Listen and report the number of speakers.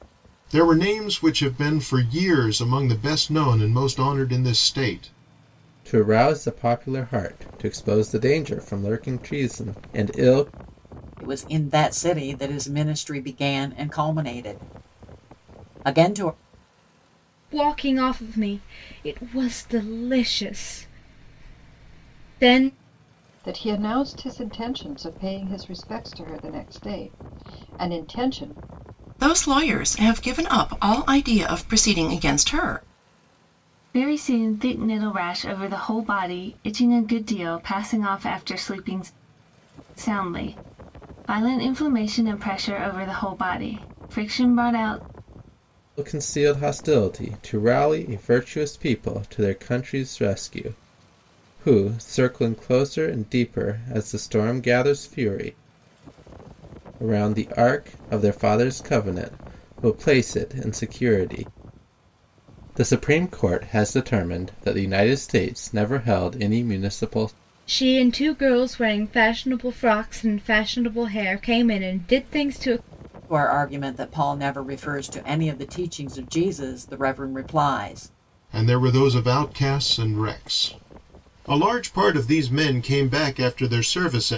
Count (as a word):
seven